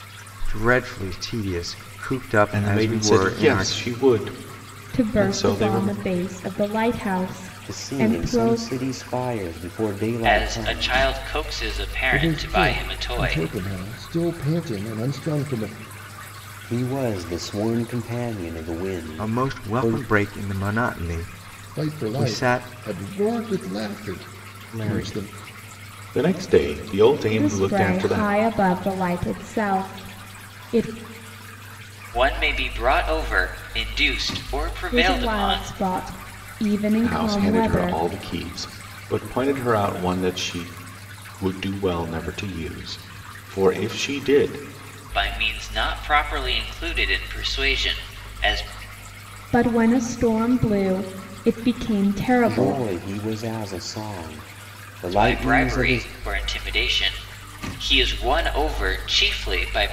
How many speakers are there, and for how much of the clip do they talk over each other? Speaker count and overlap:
6, about 20%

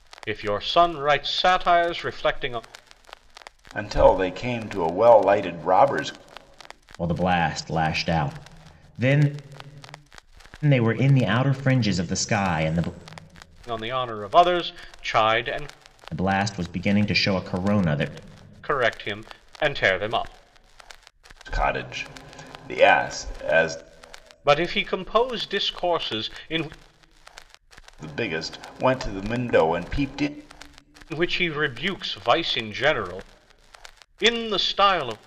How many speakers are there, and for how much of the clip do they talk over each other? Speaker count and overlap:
3, no overlap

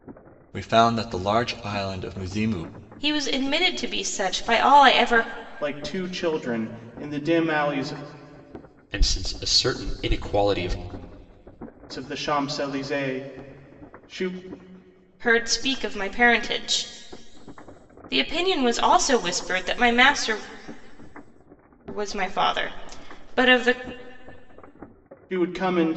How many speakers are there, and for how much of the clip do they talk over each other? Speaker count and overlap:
4, no overlap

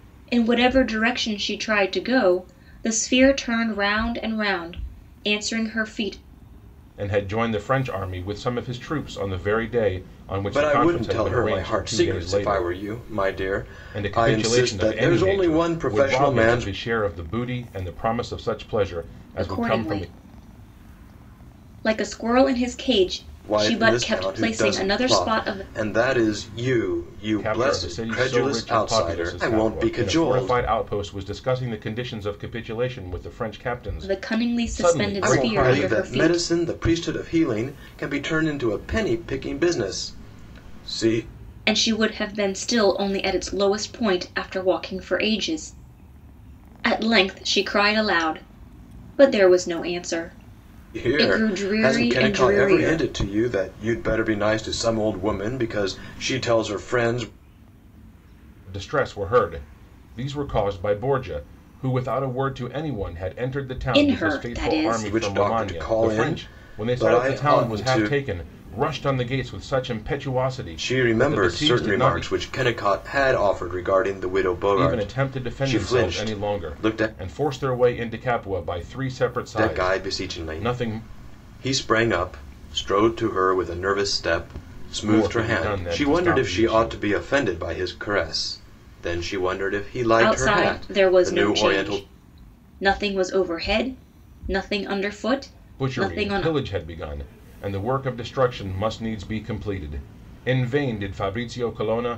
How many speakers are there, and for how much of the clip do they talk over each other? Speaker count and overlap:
3, about 29%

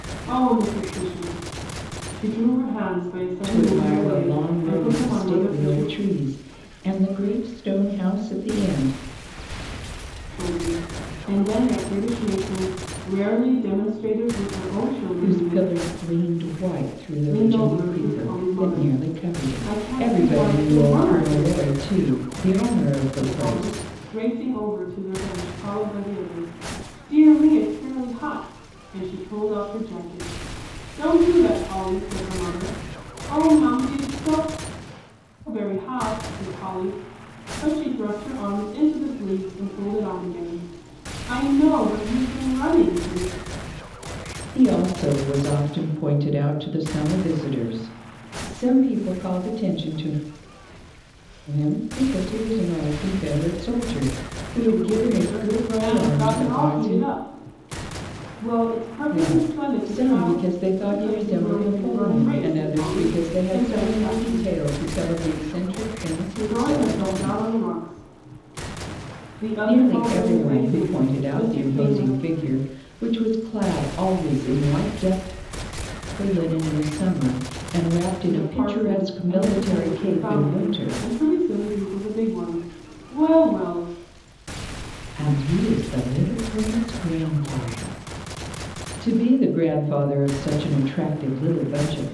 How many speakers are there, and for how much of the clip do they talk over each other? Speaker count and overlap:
2, about 24%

